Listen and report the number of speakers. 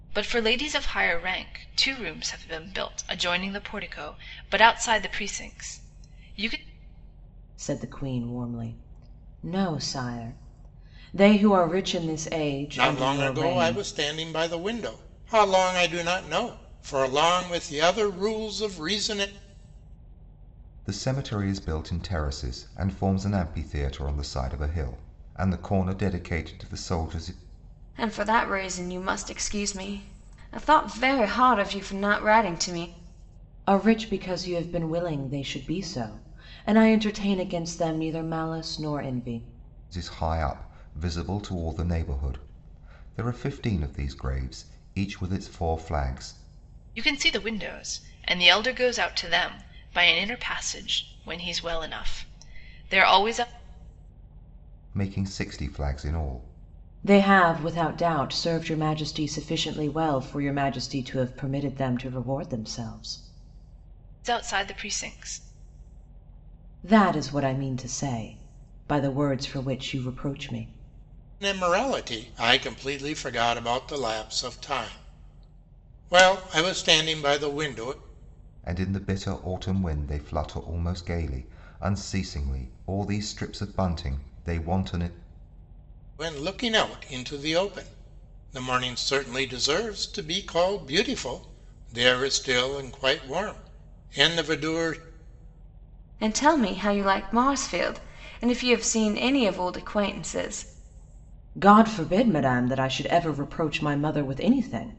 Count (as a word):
five